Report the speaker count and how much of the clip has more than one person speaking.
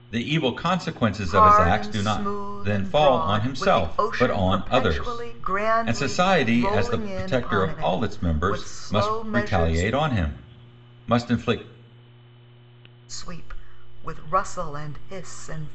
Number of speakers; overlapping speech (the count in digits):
2, about 53%